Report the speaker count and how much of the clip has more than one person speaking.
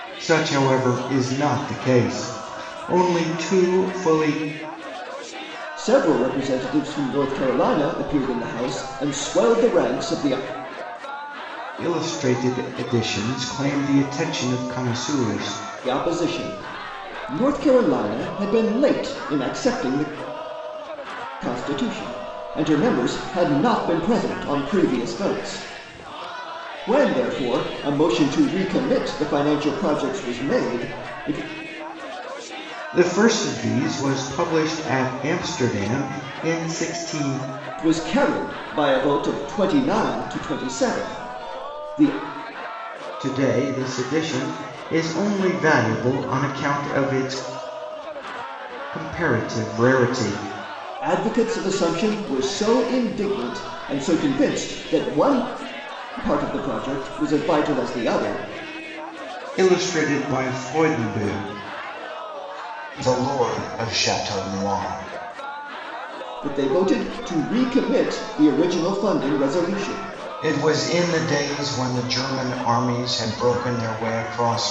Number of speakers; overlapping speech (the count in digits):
2, no overlap